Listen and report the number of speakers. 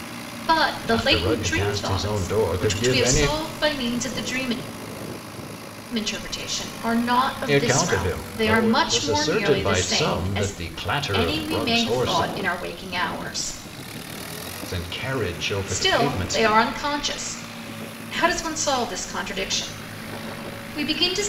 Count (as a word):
two